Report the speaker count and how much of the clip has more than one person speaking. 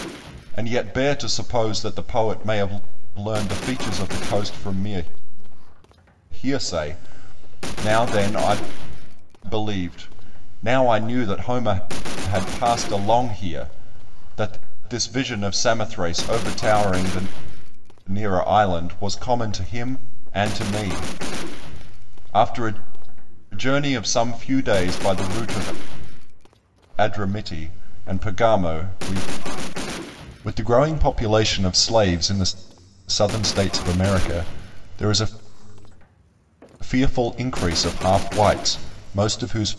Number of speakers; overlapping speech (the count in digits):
1, no overlap